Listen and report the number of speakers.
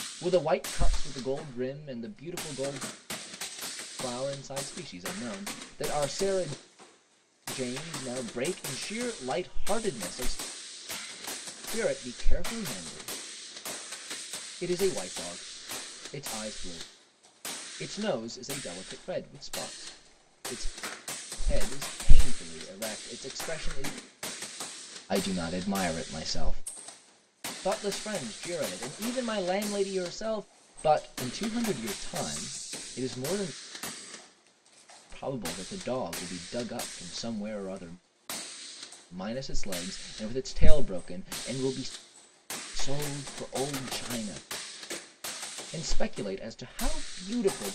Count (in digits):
1